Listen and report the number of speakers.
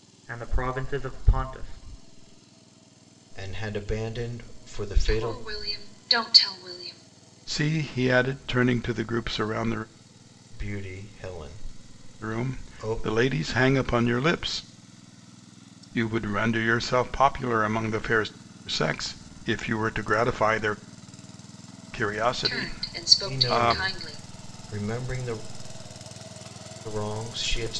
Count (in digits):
4